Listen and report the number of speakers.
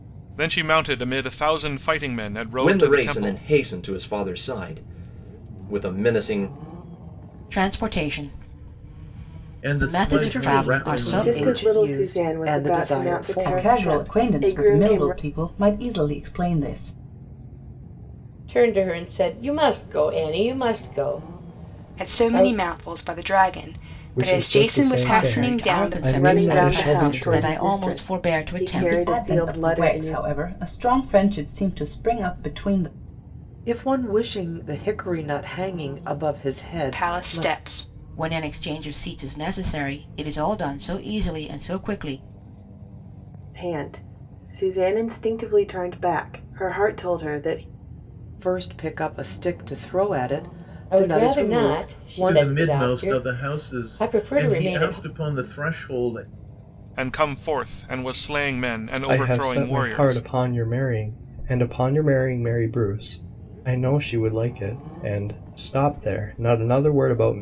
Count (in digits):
10